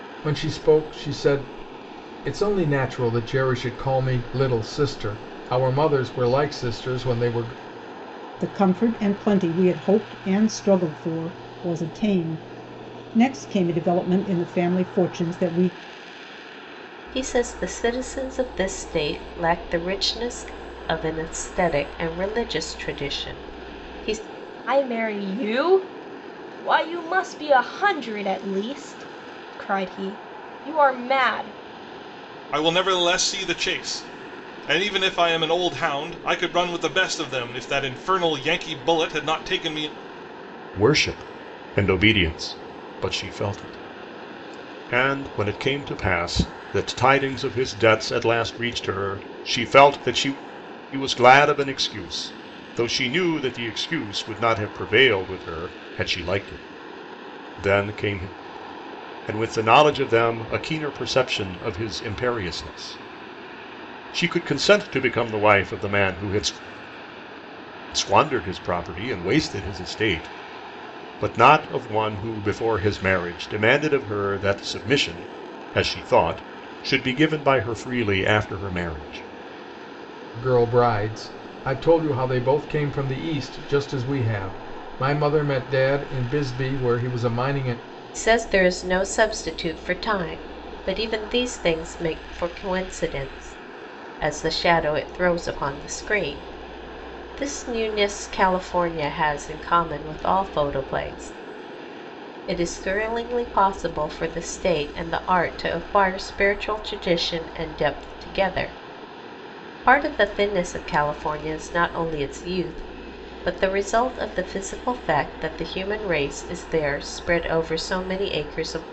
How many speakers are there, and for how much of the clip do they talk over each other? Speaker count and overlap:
6, no overlap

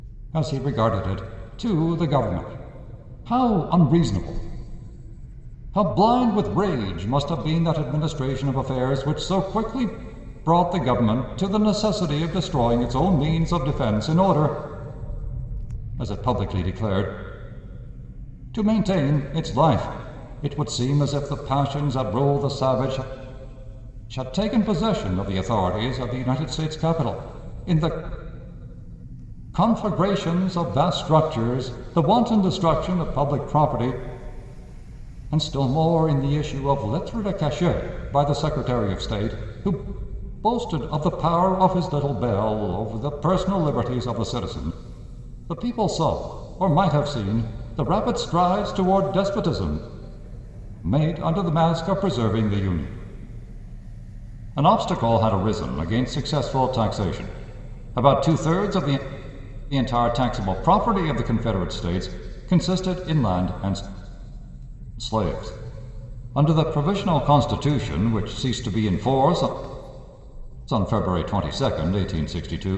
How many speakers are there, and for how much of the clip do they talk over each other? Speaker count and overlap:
1, no overlap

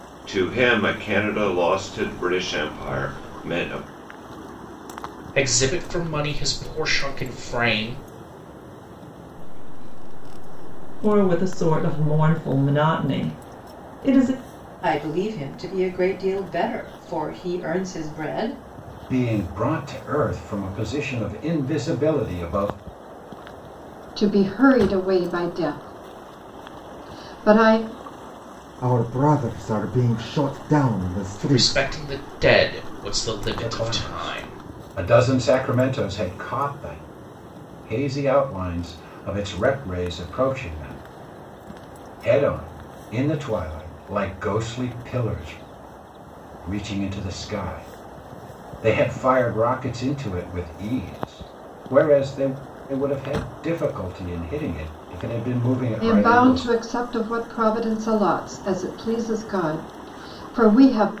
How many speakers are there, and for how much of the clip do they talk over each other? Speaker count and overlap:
8, about 6%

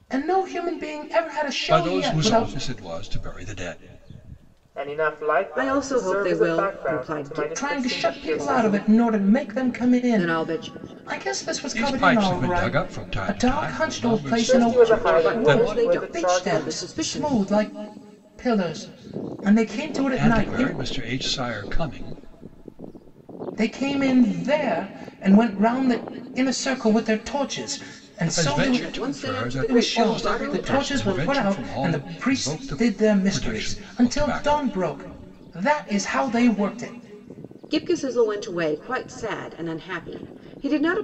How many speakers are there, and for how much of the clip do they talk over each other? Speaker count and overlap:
4, about 45%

